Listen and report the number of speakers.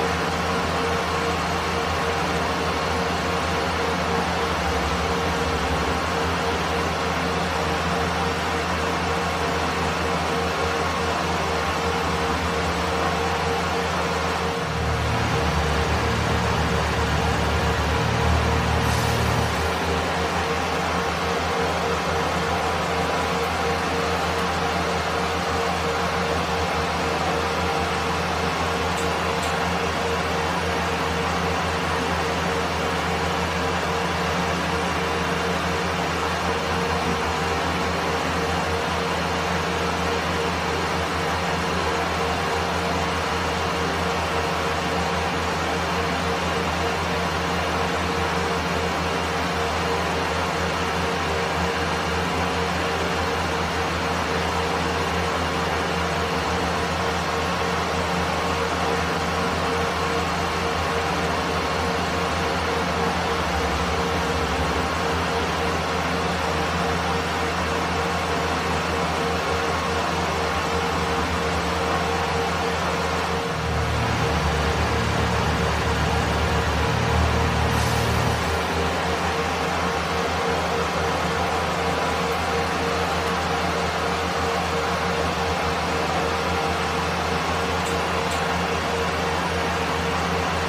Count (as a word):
zero